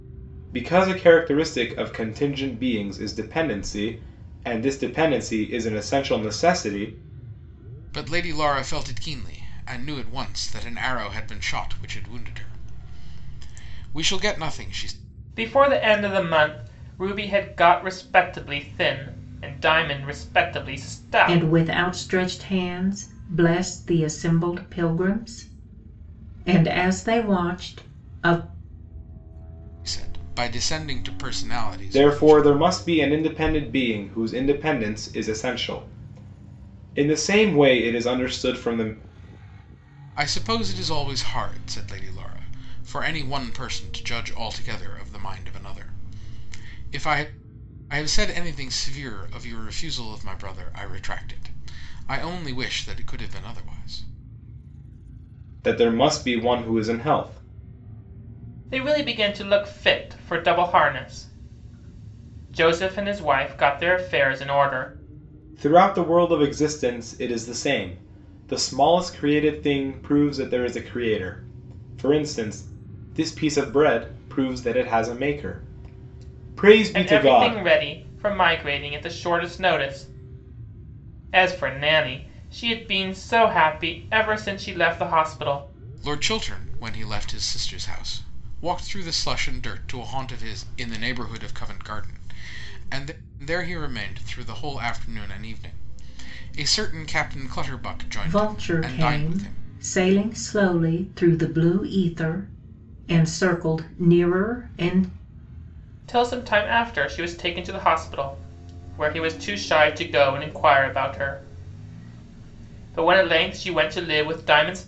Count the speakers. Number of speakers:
four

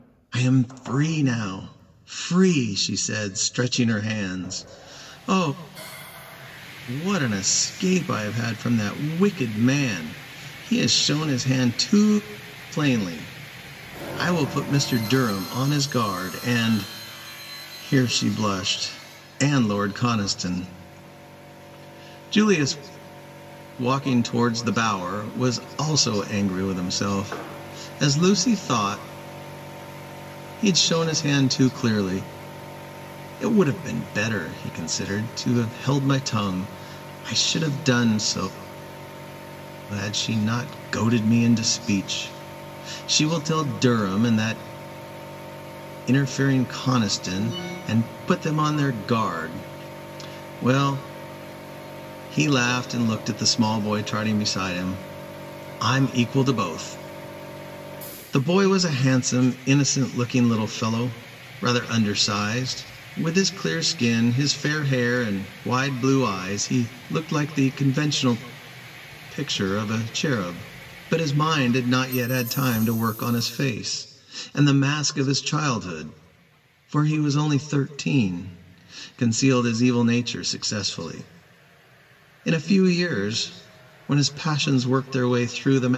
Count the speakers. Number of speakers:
one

